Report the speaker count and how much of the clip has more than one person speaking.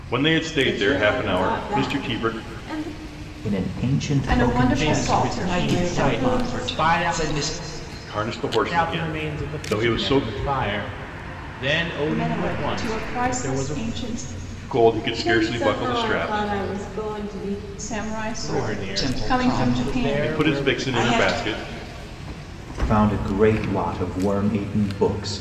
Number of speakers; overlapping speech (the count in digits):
6, about 48%